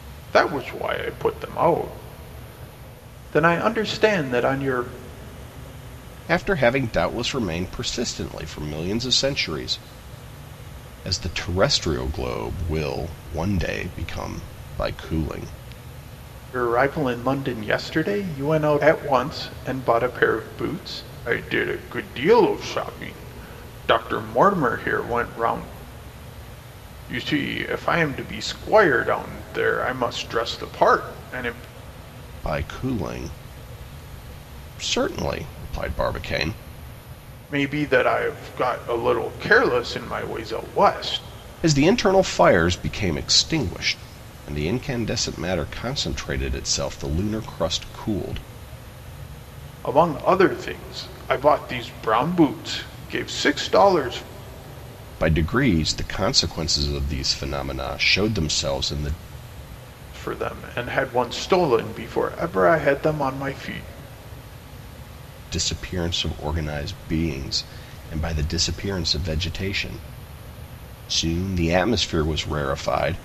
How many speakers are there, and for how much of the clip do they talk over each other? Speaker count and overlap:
2, no overlap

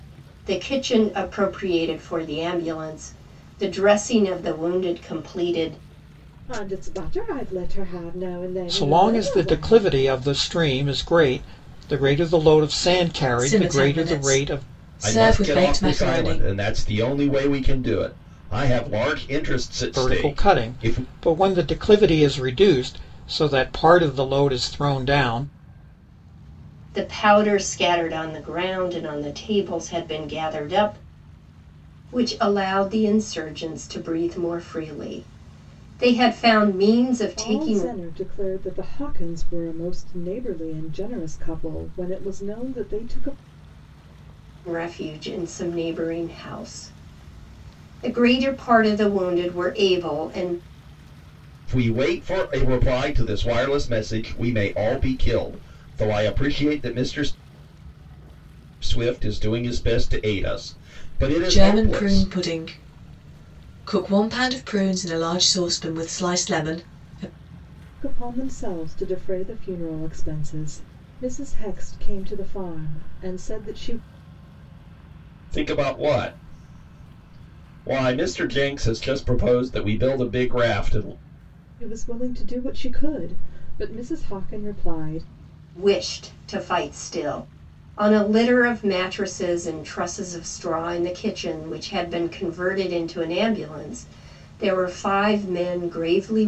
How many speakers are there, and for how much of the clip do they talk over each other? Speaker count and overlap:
5, about 7%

